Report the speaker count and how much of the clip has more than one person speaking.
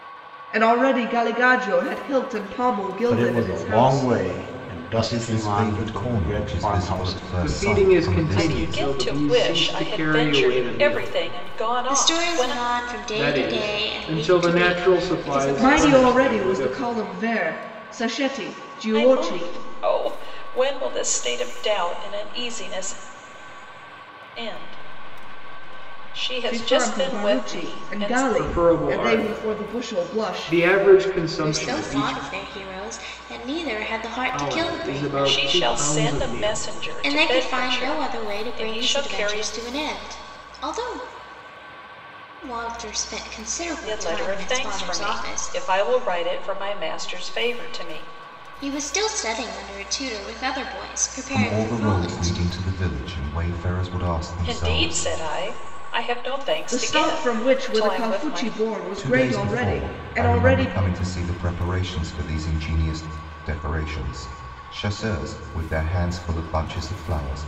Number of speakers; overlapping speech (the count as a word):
six, about 44%